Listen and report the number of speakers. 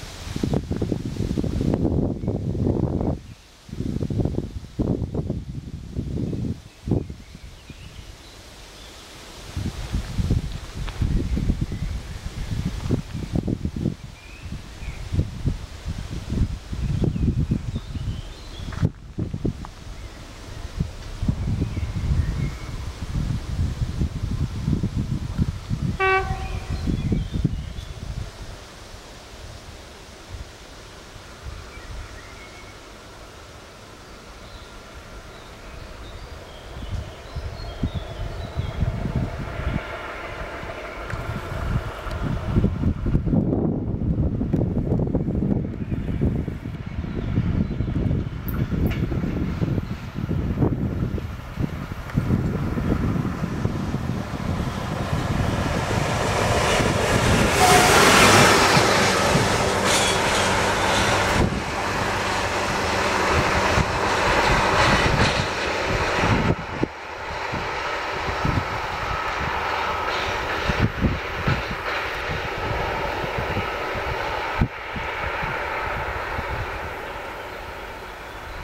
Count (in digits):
0